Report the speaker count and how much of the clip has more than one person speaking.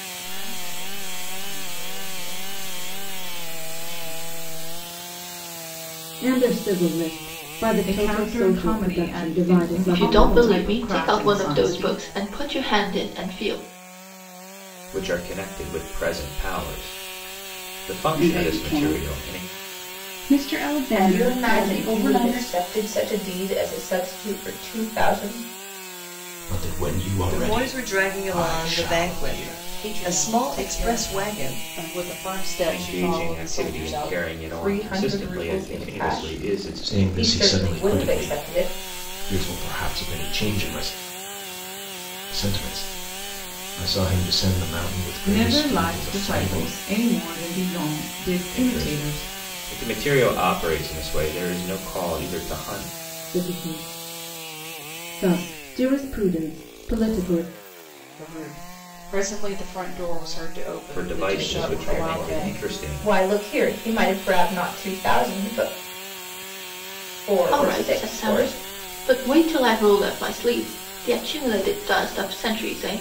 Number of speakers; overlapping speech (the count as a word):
ten, about 32%